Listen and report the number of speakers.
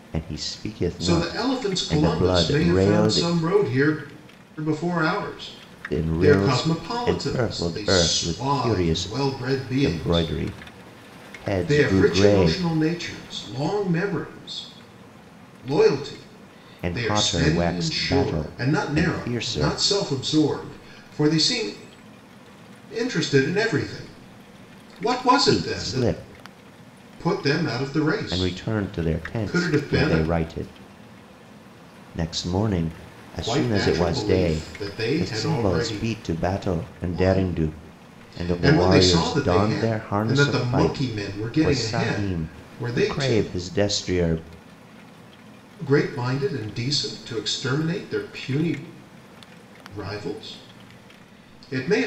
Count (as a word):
two